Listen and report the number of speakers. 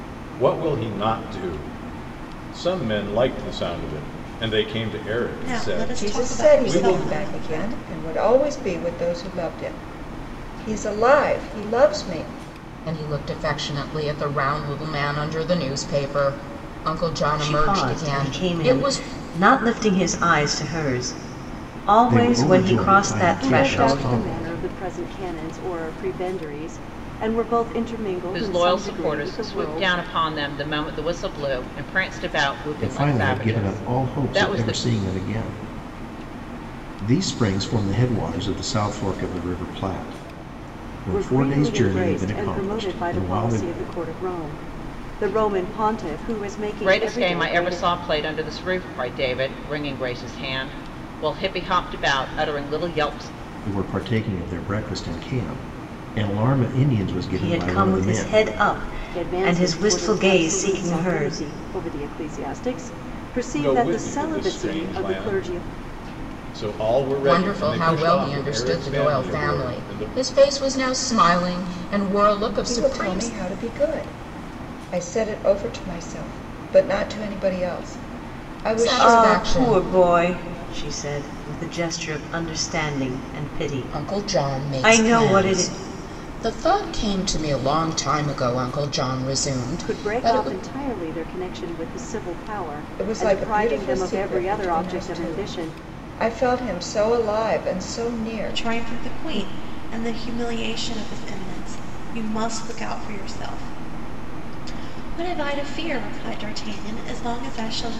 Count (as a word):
eight